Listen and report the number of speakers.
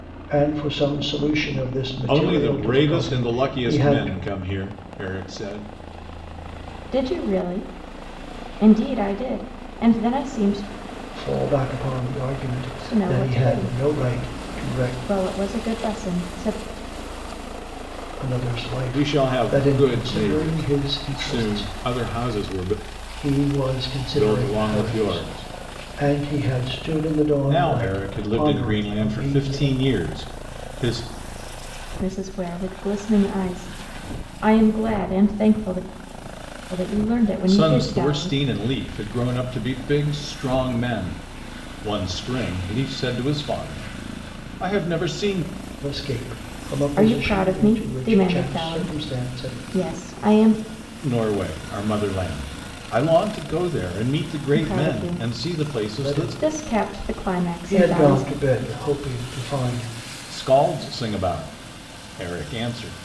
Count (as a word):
three